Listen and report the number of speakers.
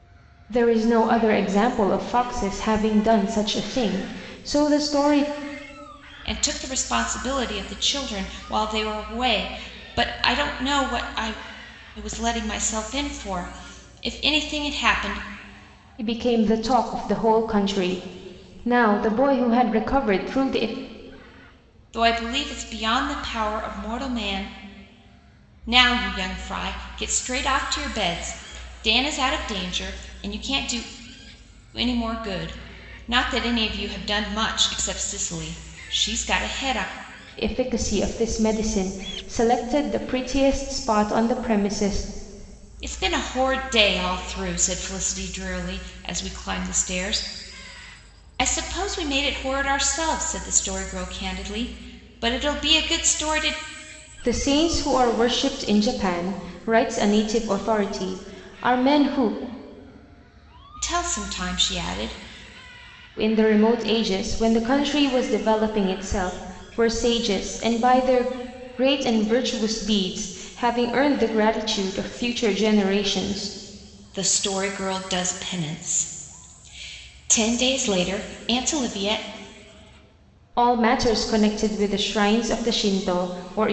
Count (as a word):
two